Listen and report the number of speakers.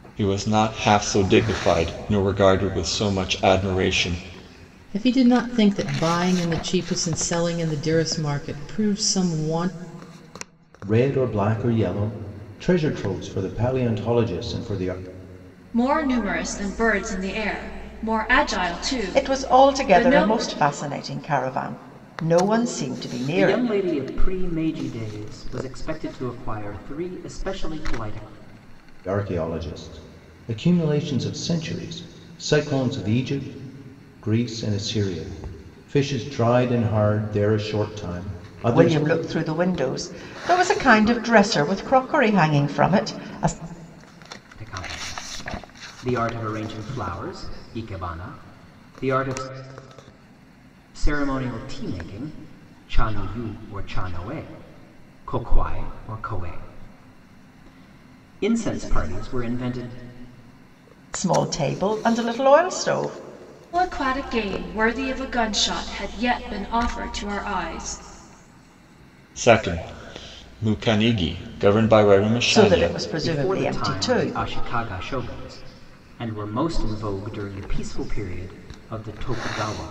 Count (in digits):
6